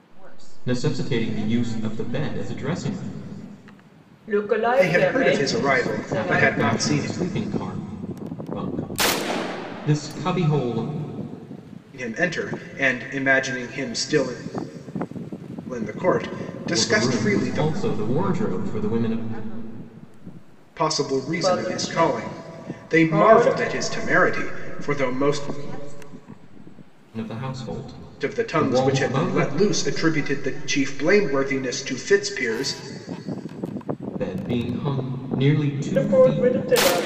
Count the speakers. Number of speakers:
4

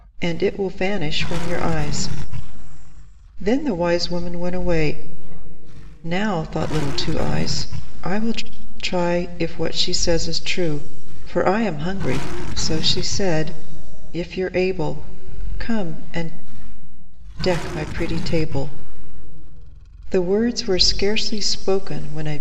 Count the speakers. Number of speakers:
1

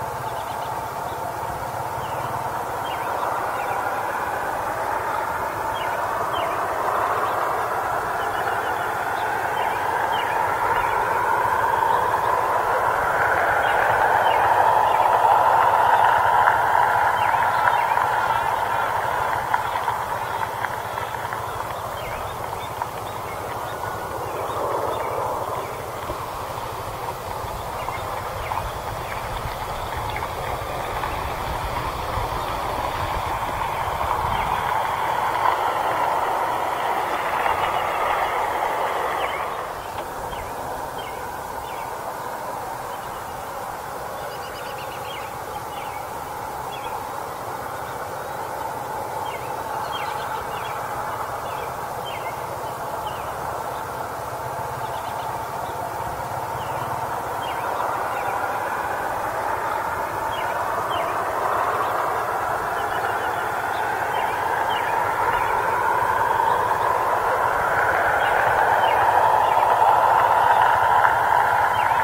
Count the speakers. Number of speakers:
0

